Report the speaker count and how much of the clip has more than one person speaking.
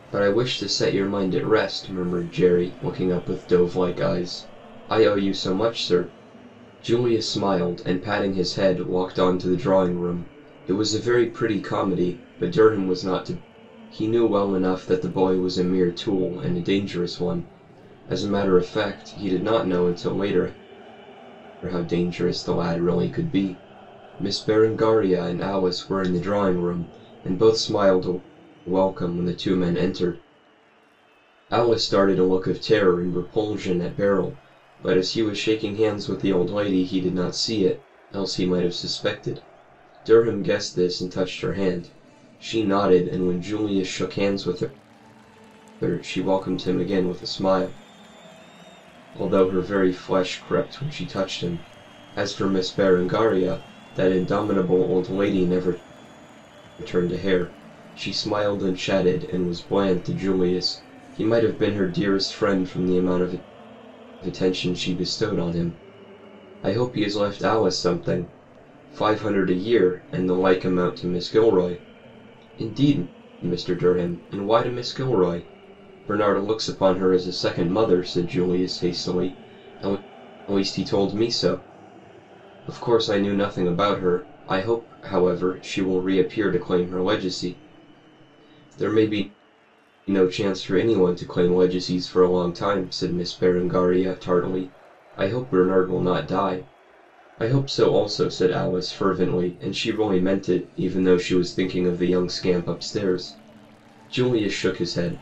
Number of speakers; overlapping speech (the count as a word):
one, no overlap